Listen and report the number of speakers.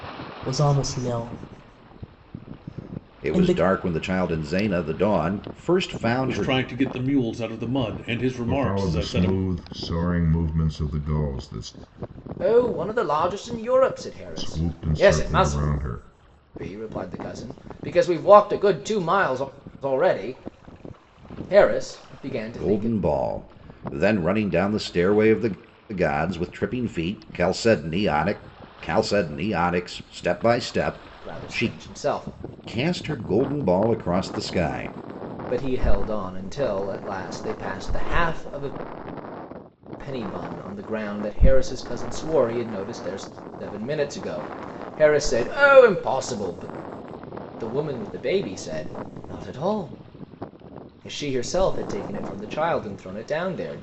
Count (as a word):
five